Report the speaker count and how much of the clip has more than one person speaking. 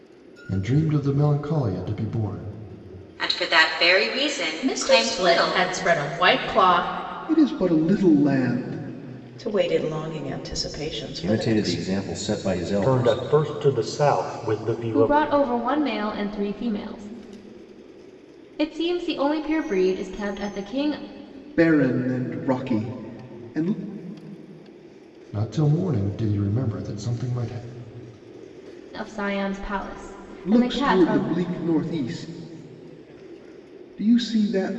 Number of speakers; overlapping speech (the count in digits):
8, about 10%